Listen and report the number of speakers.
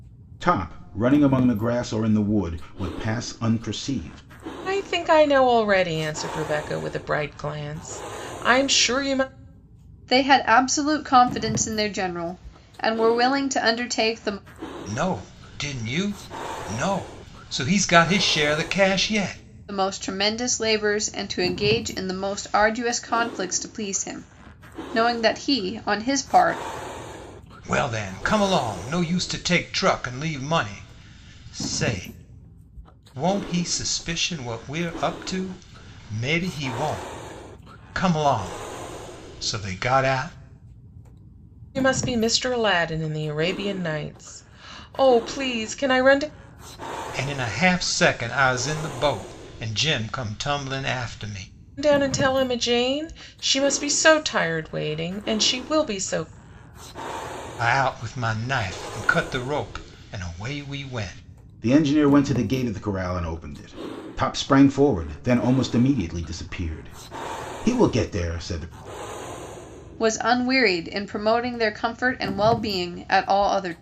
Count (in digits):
4